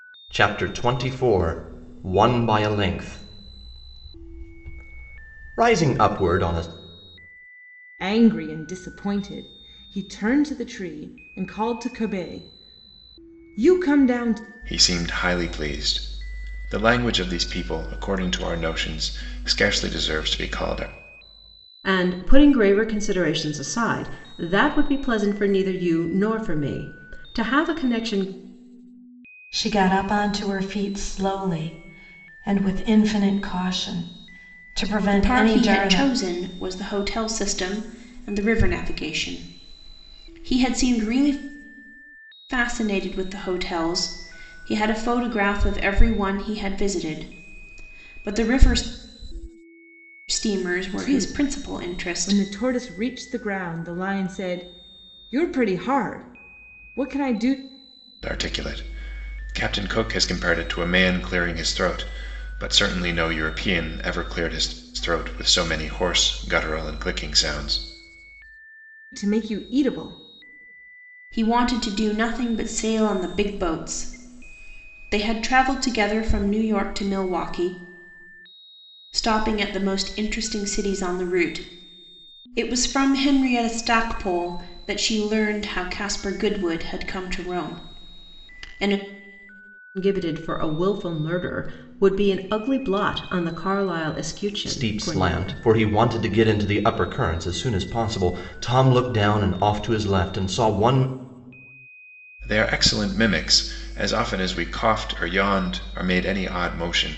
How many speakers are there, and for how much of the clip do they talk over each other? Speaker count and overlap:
six, about 3%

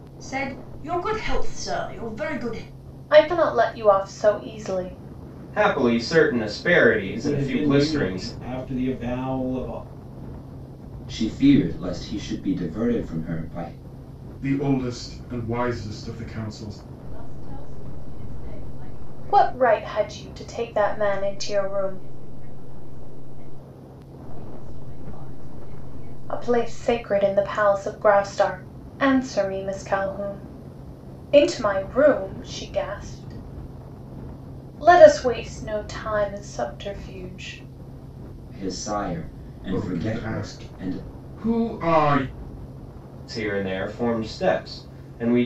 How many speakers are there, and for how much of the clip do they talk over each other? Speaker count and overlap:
seven, about 11%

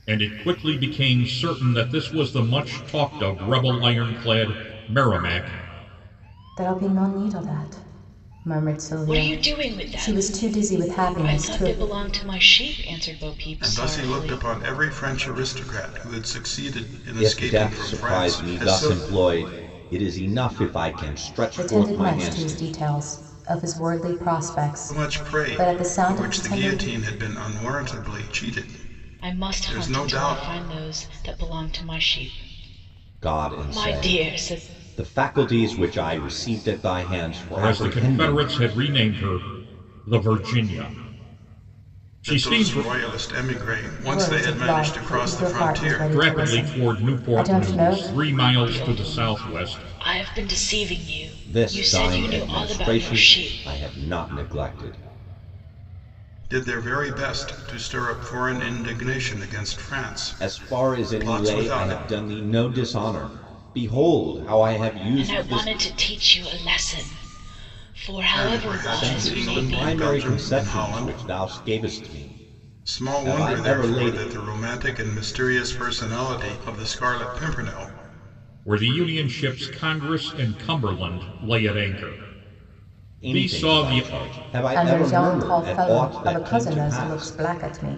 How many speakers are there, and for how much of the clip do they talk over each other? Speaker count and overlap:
five, about 34%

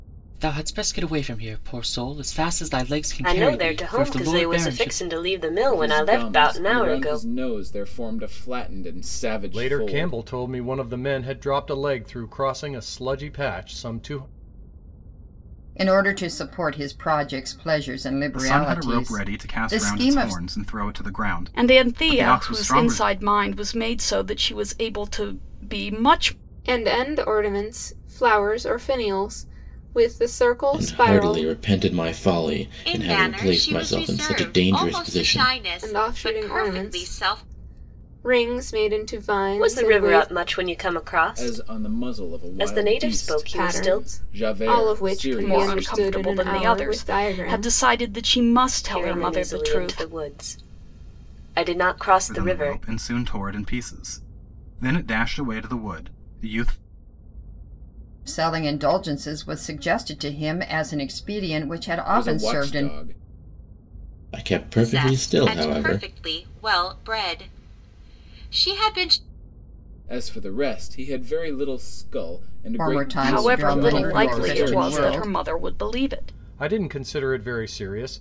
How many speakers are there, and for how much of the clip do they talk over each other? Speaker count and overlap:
ten, about 36%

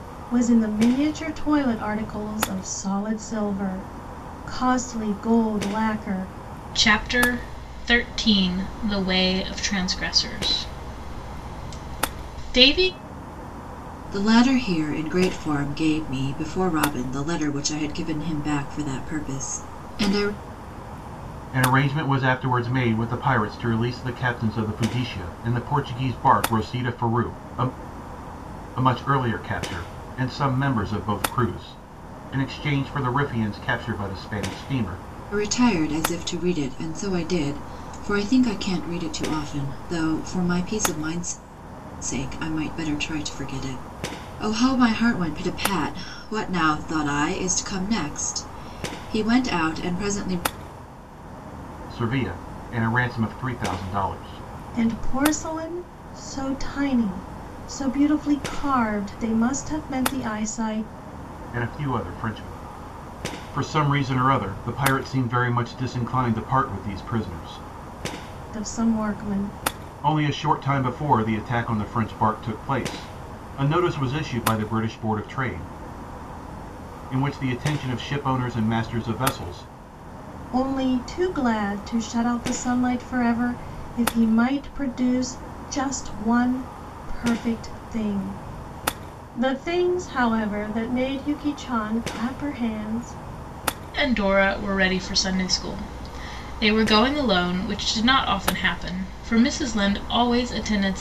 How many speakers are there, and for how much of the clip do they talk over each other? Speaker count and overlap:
four, no overlap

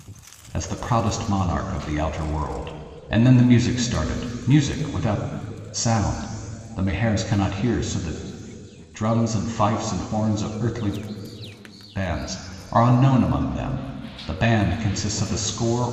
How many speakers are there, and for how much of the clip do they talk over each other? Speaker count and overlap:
one, no overlap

